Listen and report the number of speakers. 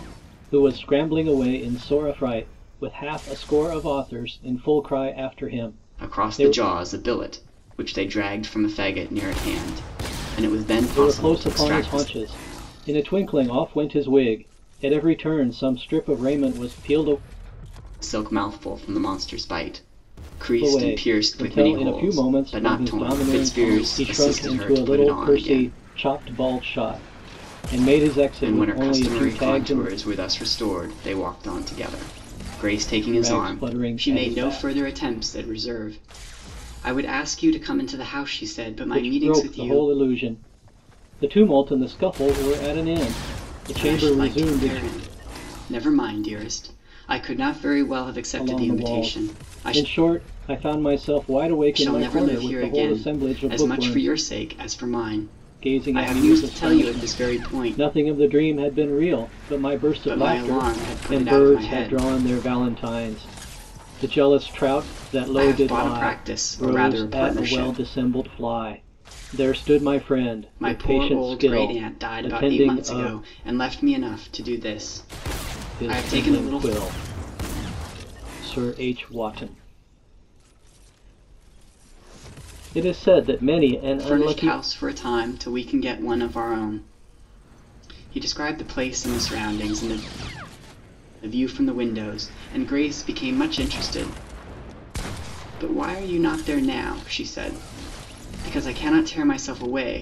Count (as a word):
two